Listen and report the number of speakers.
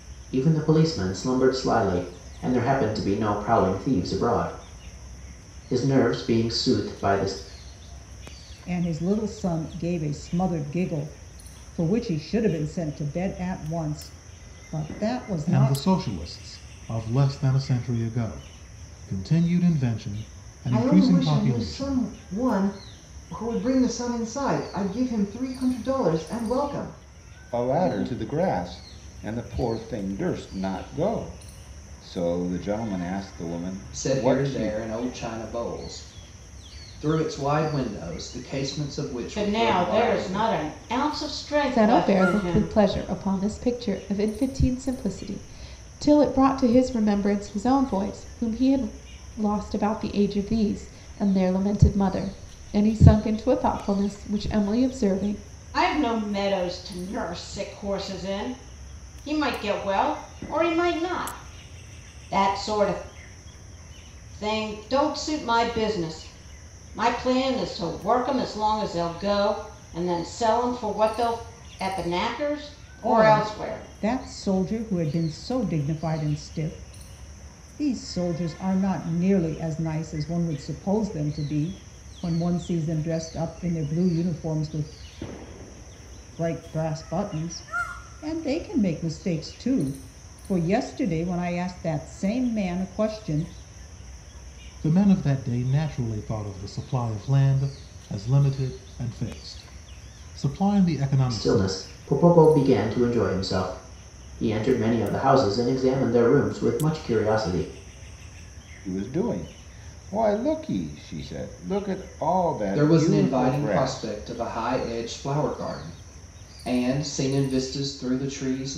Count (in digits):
8